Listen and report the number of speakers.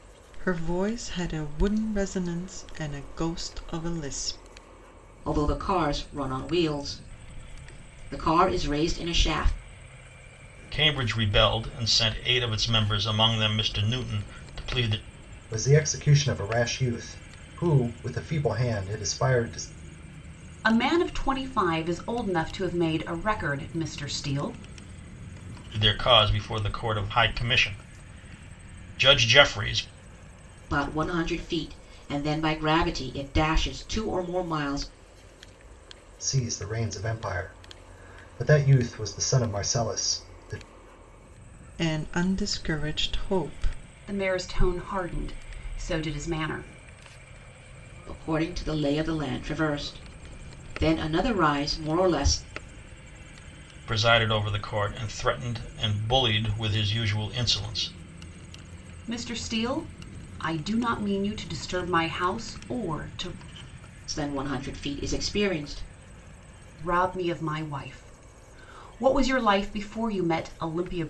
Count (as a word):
five